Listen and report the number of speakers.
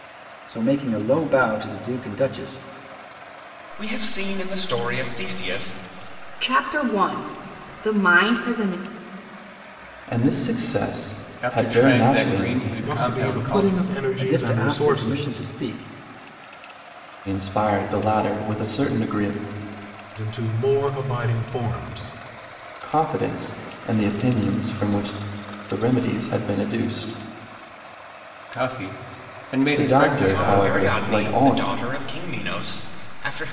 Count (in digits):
6